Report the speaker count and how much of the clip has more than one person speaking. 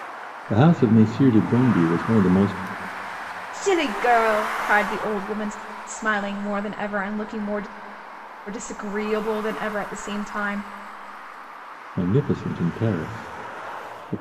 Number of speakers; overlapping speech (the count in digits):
2, no overlap